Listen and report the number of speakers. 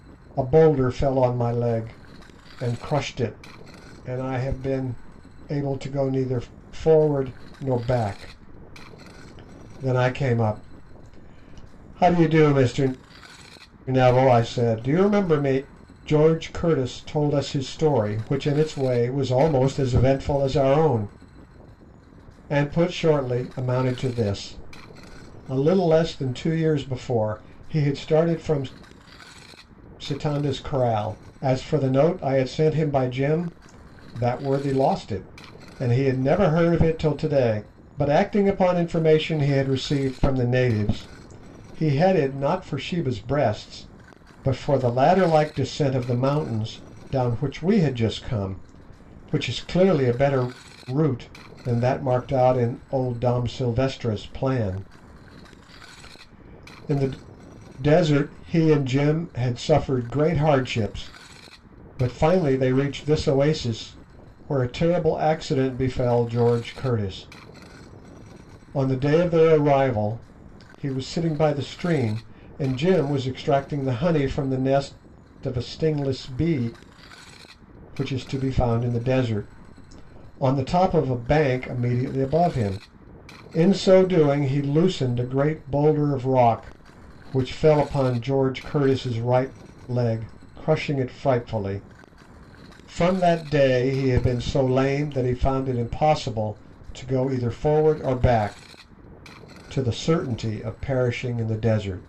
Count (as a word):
one